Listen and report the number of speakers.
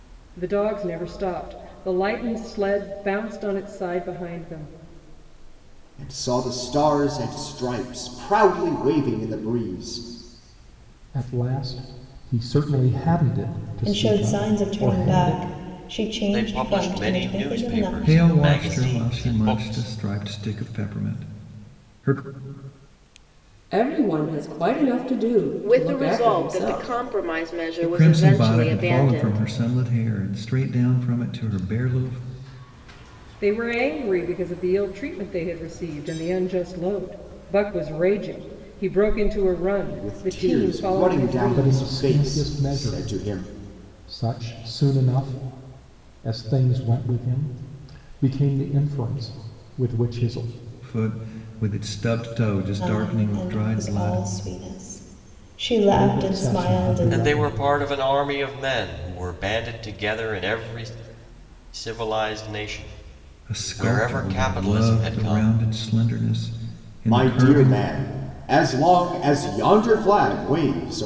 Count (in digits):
8